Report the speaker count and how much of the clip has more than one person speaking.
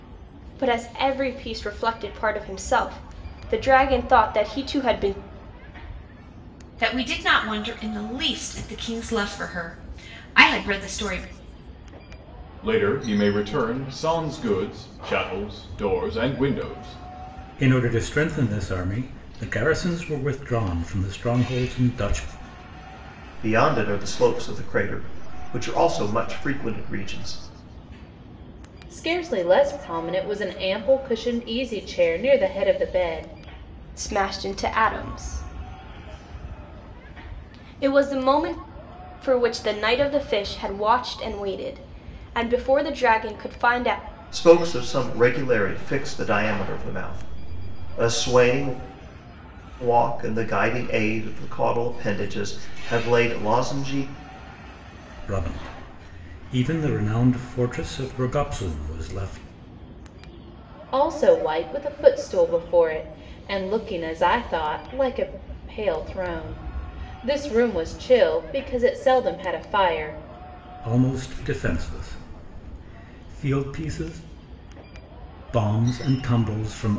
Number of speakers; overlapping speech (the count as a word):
six, no overlap